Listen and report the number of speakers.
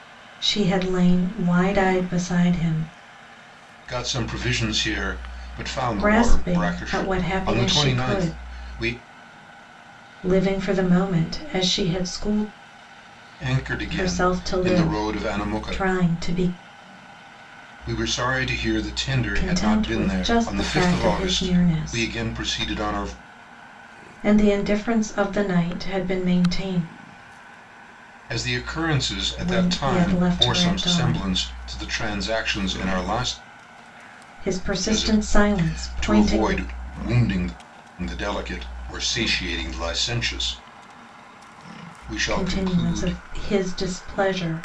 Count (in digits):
2